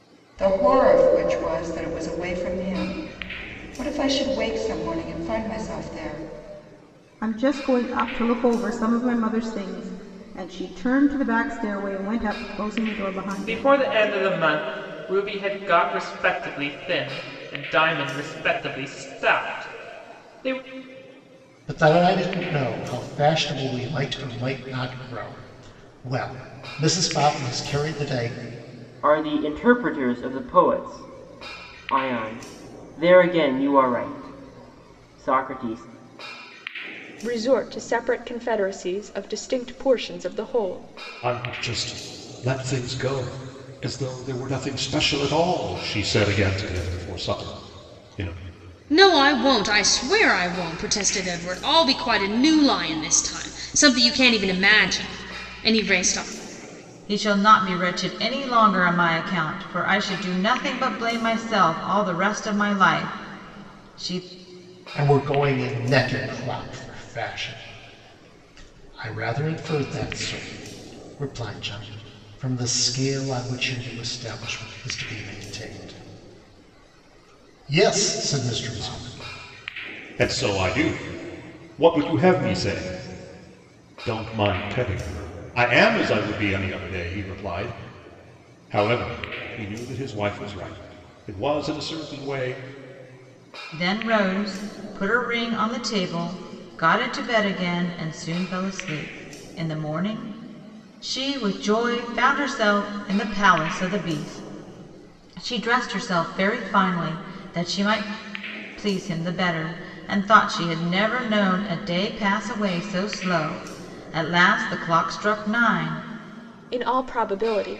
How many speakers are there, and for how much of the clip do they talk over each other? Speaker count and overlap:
9, about 1%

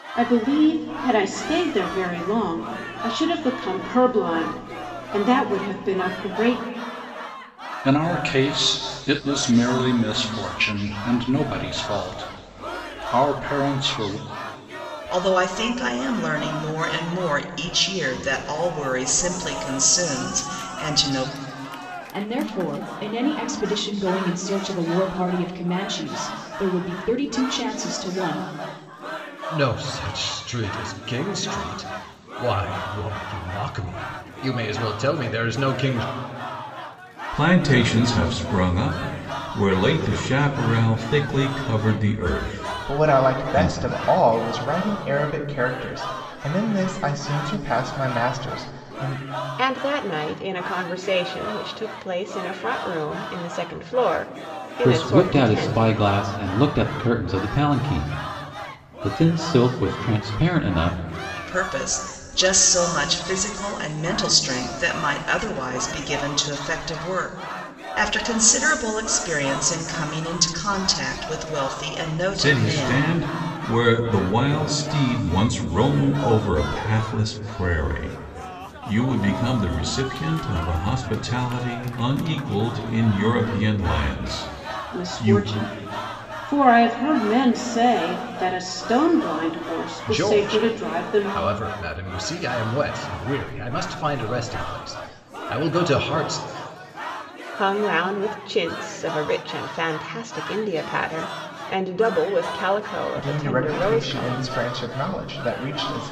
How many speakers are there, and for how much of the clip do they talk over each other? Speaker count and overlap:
9, about 6%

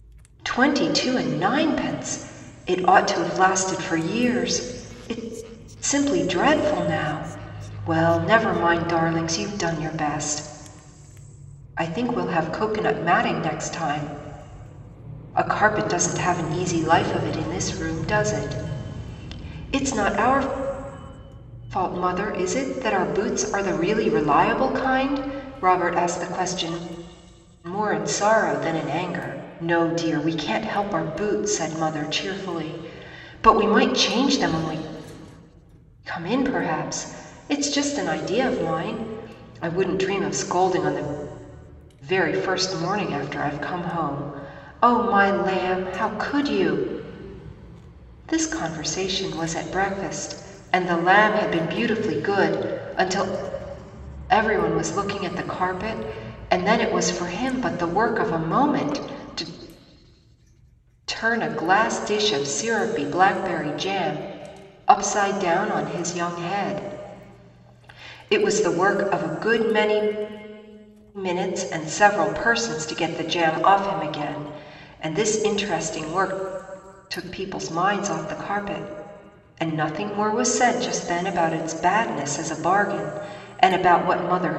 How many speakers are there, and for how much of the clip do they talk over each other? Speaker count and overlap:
1, no overlap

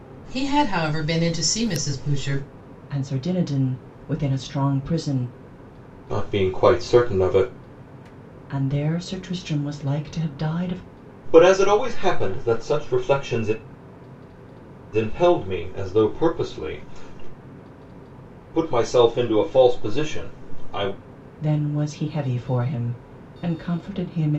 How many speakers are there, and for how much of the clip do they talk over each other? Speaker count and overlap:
3, no overlap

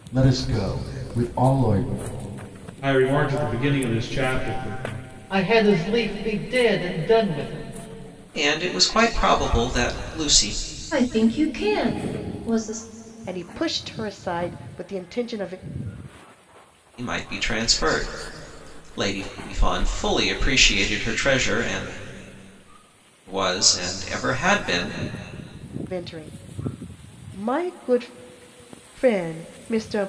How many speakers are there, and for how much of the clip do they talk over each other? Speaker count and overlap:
6, no overlap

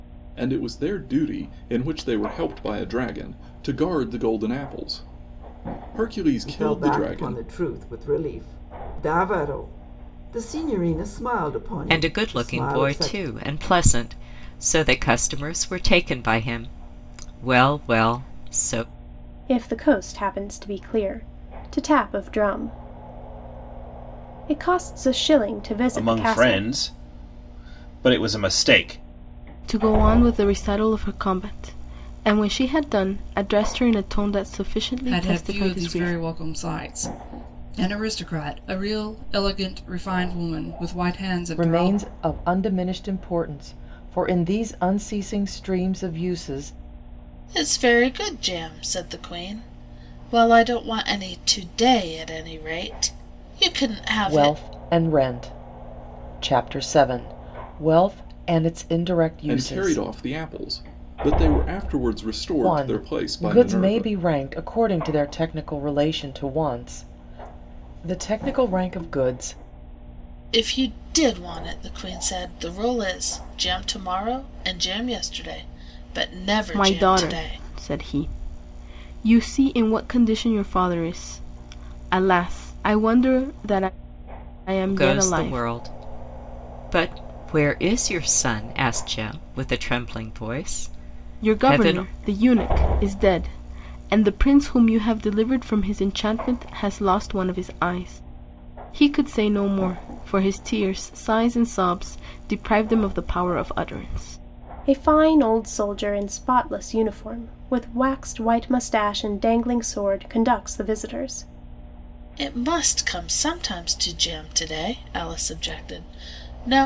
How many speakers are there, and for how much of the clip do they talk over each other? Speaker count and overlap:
9, about 8%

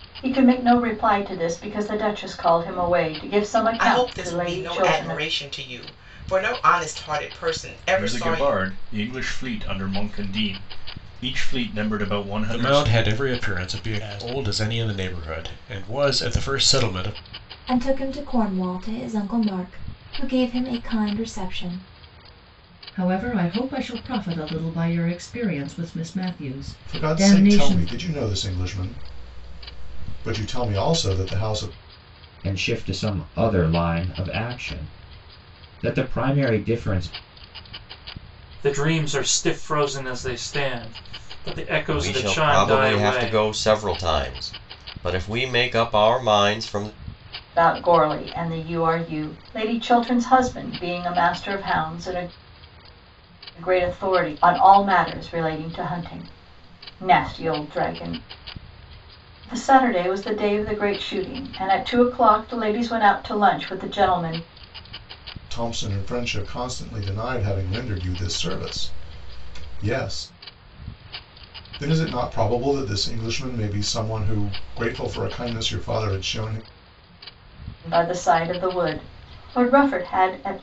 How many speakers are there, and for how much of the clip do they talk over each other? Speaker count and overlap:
10, about 6%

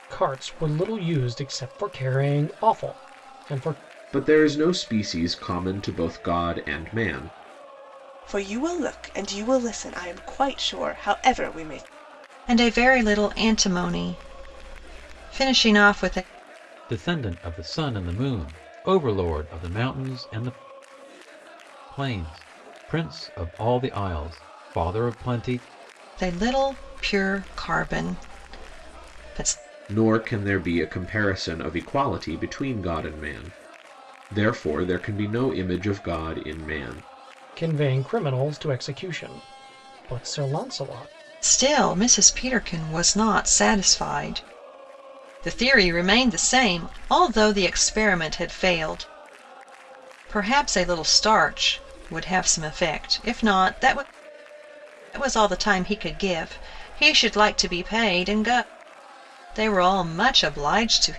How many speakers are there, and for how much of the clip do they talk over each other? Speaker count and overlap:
5, no overlap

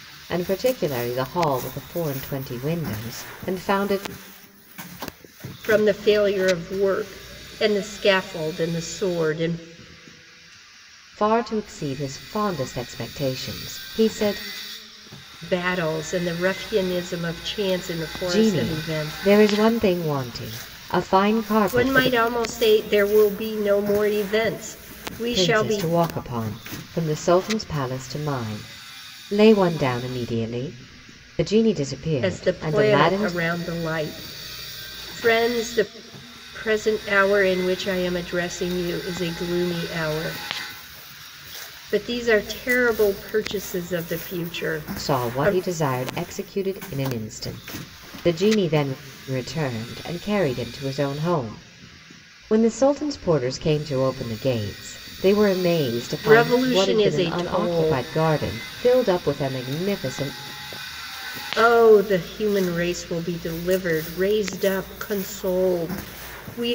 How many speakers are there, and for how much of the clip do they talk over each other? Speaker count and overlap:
2, about 8%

